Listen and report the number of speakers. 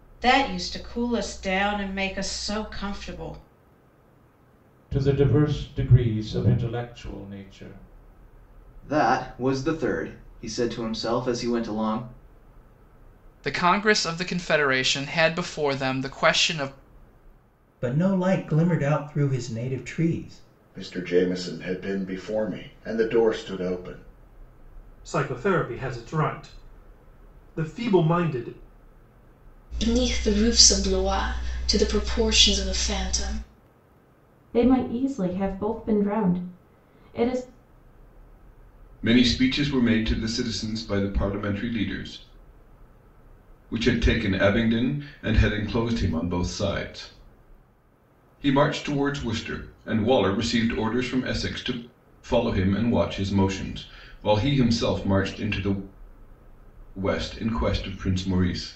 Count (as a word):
ten